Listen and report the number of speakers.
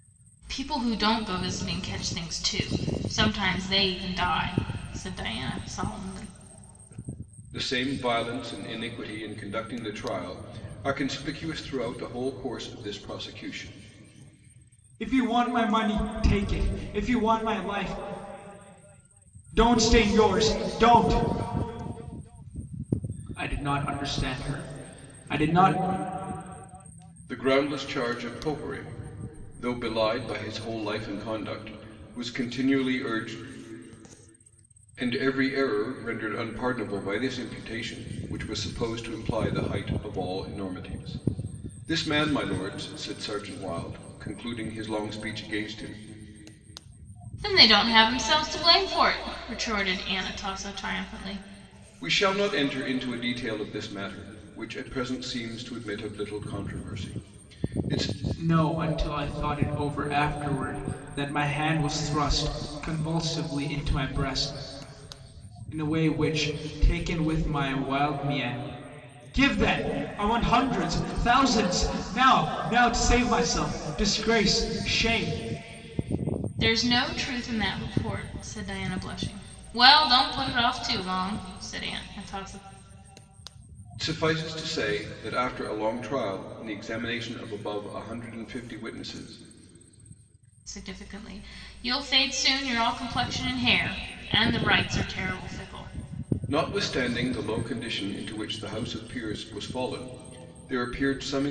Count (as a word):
three